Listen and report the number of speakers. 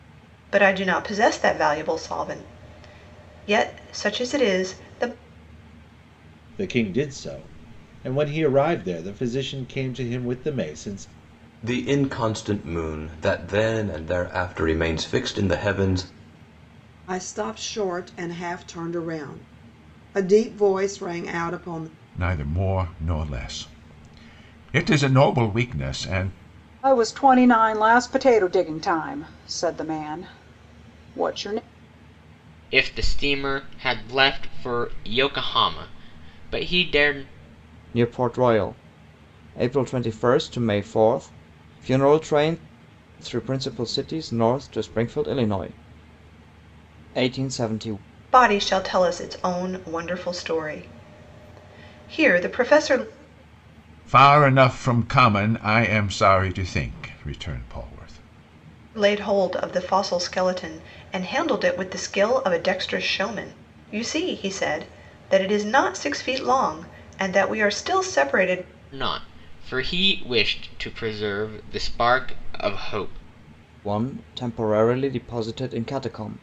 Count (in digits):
8